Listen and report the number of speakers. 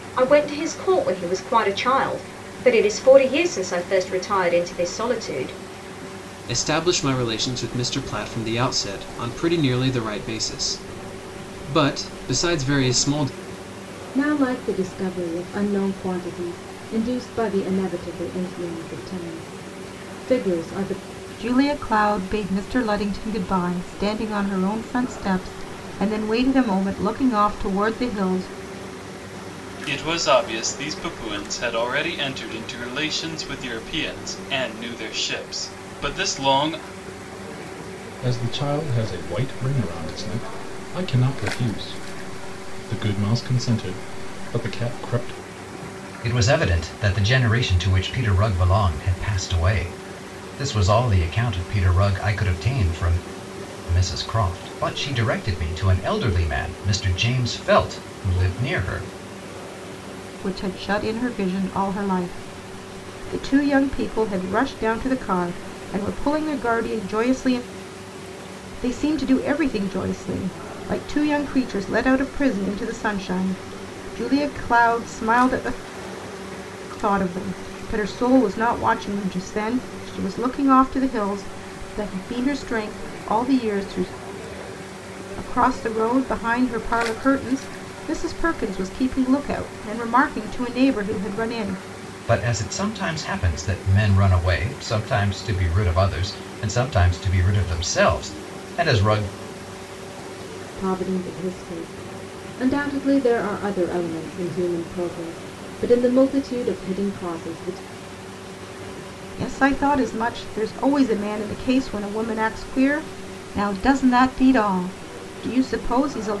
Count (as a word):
seven